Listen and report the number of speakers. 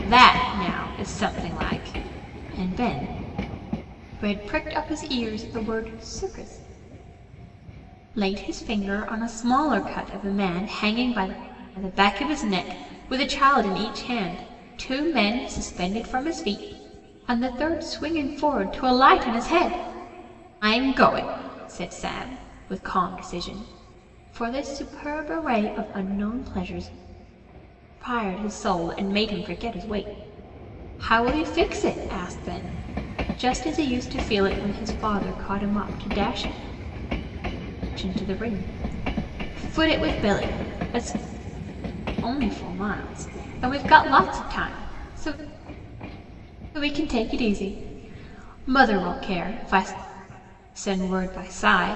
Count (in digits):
1